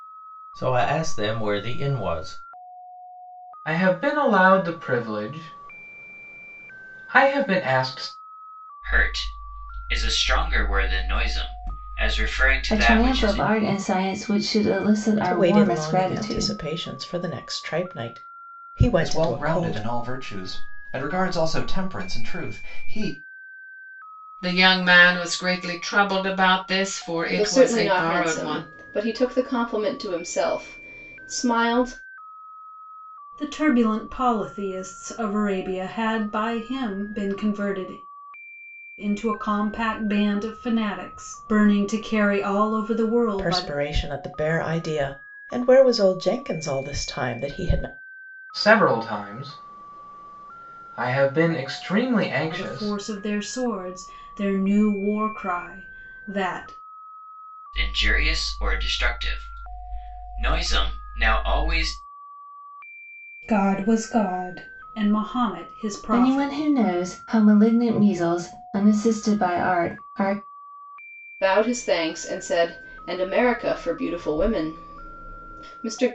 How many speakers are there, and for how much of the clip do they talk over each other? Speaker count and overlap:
nine, about 8%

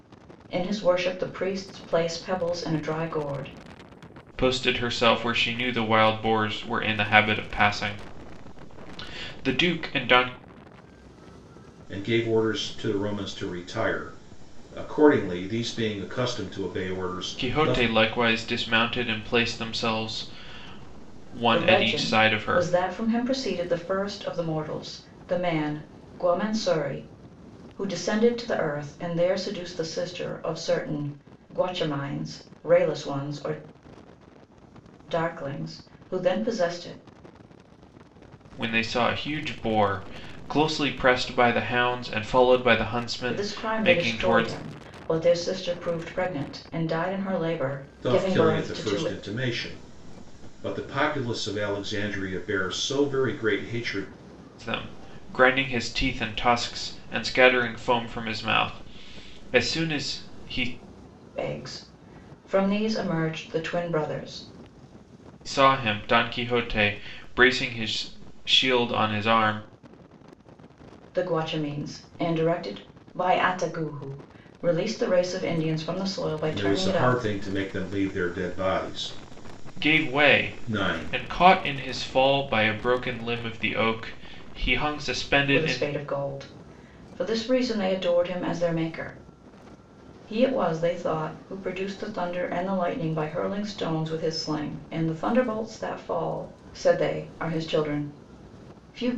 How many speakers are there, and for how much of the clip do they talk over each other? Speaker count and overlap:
three, about 7%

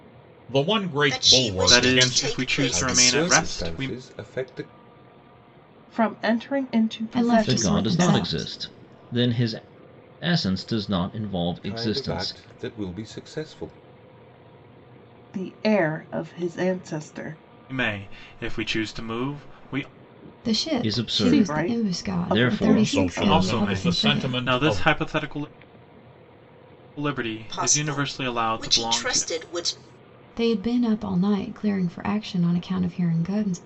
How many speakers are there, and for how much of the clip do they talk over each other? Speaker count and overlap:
seven, about 33%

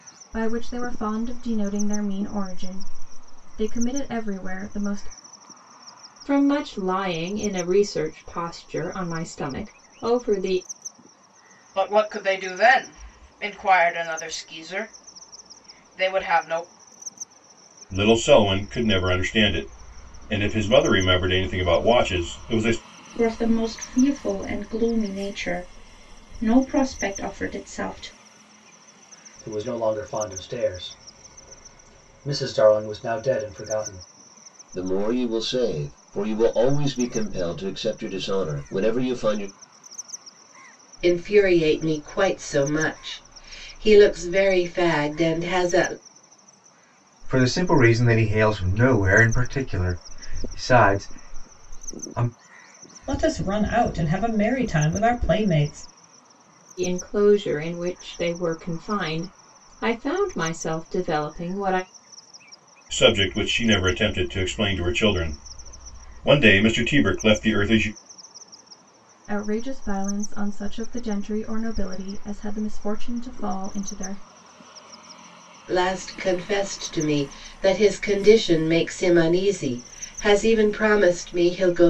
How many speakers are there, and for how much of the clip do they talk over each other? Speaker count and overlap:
ten, no overlap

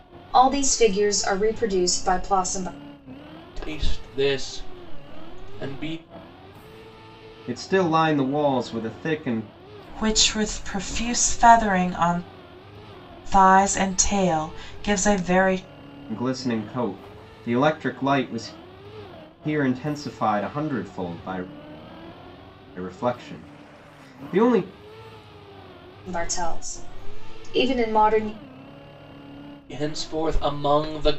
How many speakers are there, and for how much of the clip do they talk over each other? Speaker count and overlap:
four, no overlap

